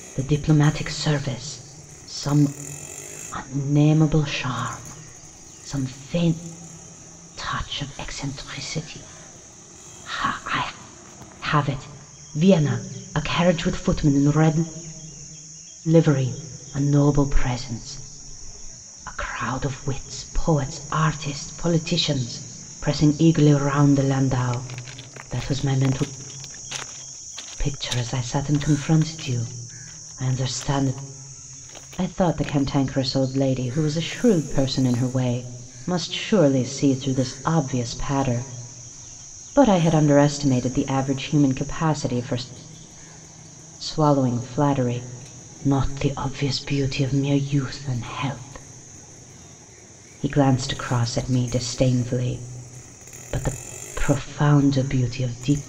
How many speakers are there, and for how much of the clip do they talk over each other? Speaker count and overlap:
1, no overlap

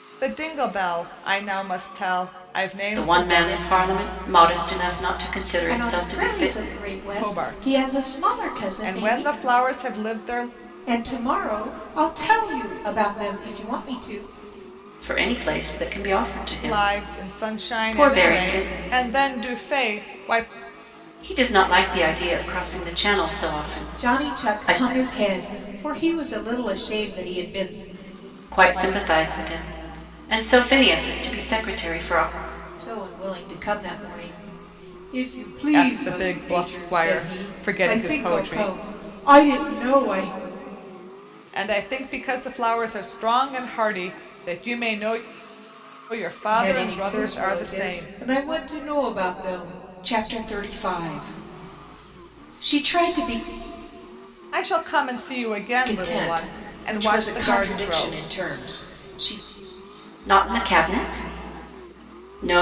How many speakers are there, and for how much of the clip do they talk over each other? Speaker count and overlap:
3, about 22%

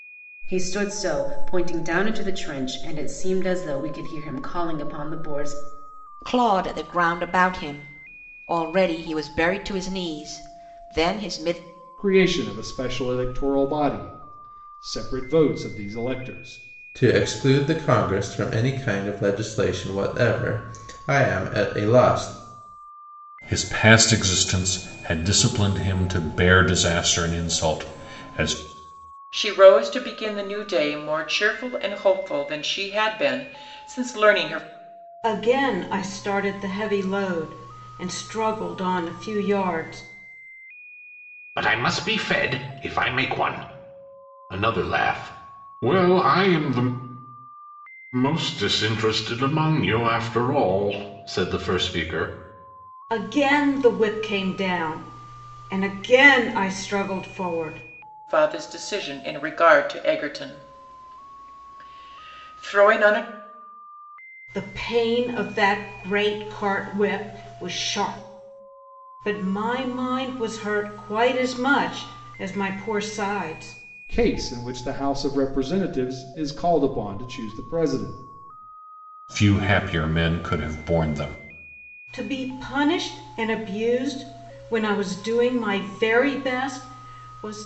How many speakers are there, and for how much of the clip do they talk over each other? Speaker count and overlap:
8, no overlap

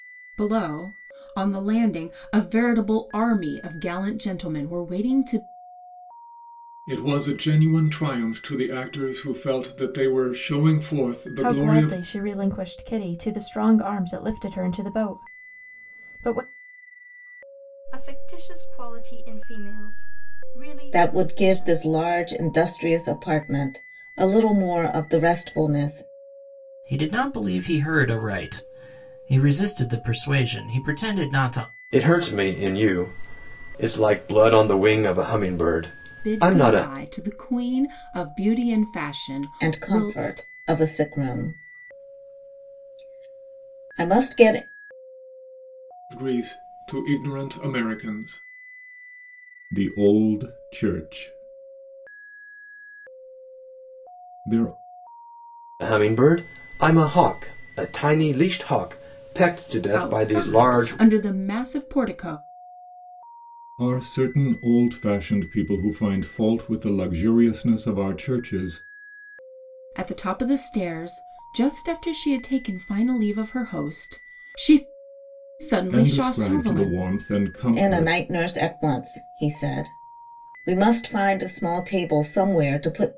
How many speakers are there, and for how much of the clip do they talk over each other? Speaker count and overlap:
7, about 7%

